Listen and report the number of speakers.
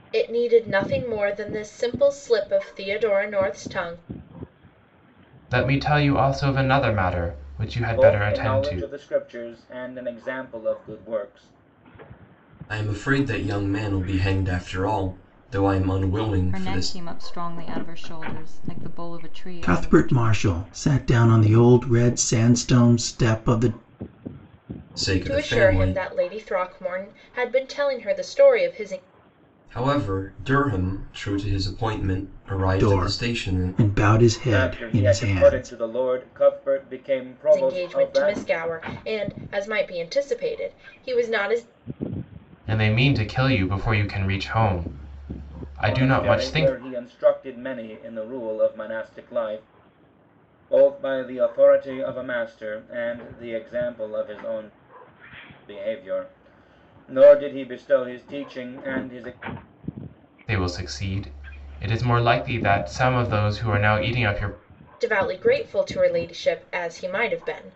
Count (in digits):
6